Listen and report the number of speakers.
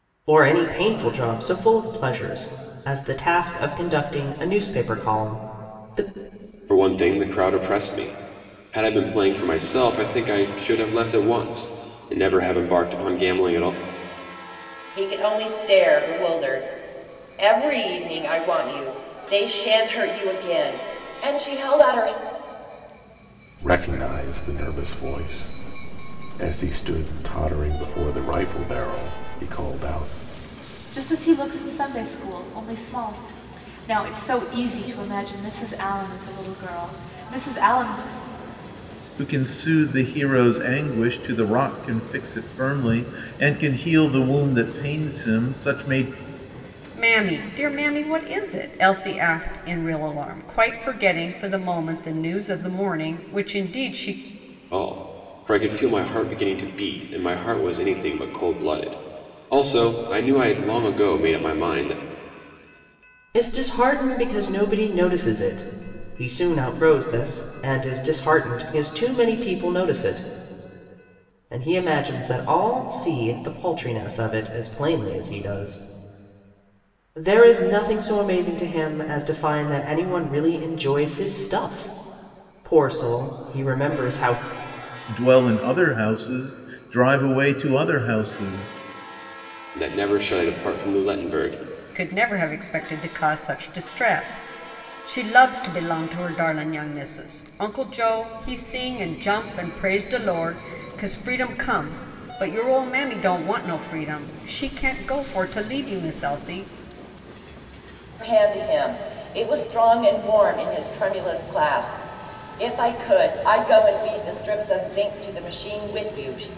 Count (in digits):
7